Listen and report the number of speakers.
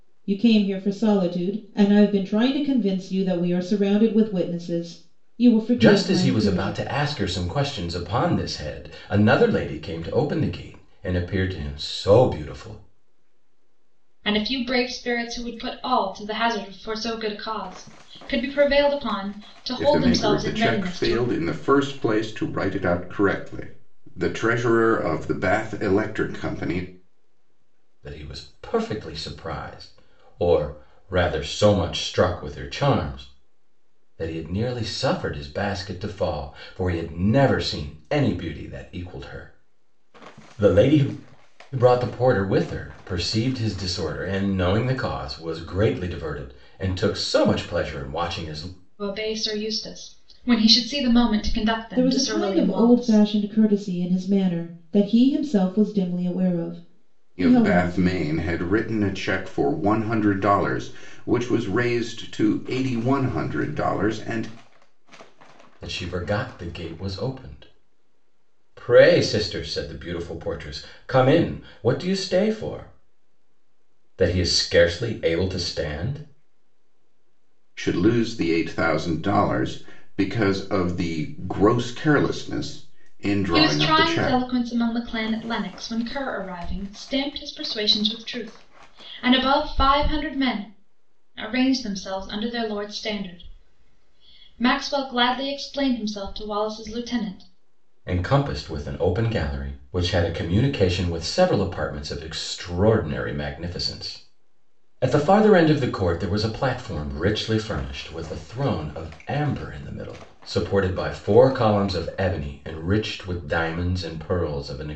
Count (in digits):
4